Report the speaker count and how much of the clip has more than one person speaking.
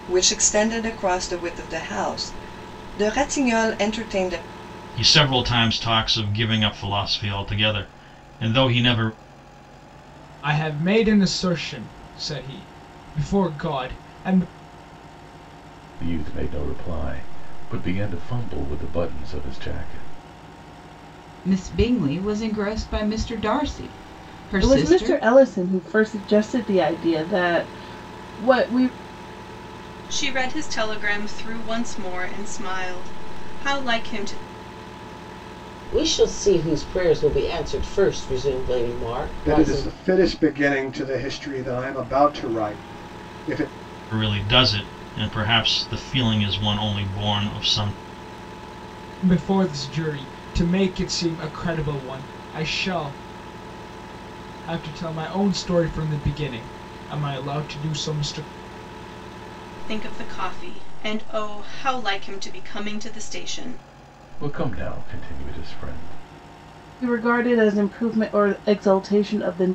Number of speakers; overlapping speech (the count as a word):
nine, about 2%